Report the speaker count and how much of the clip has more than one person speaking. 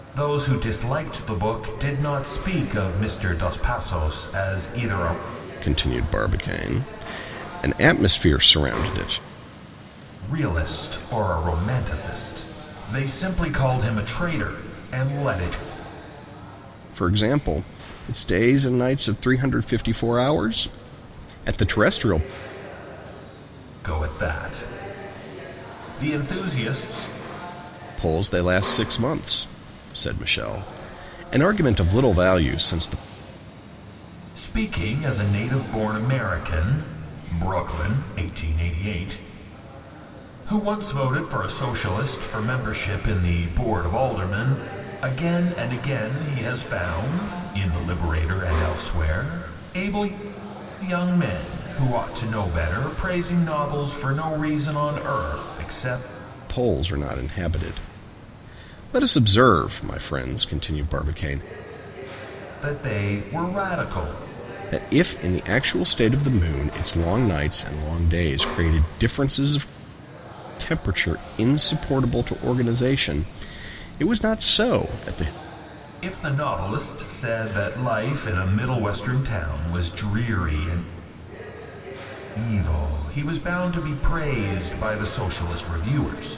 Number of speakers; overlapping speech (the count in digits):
2, no overlap